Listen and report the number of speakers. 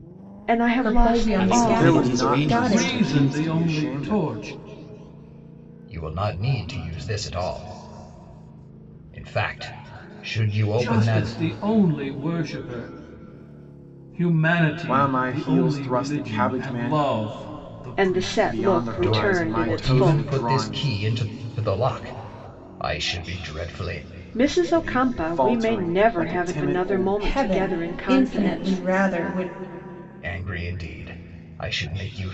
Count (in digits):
6